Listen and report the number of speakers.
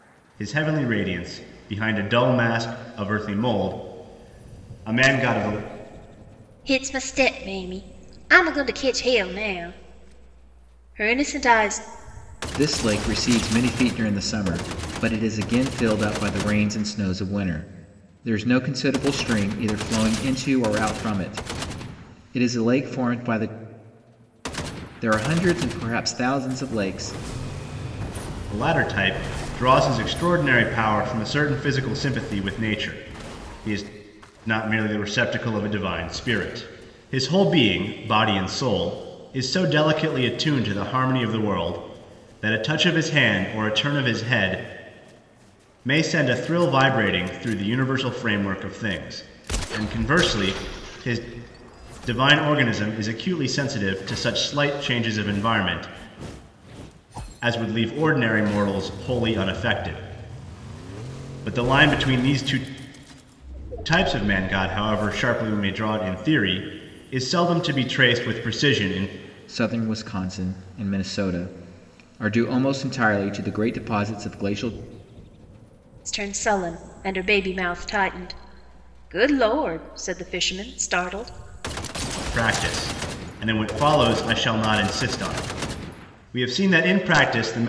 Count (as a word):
three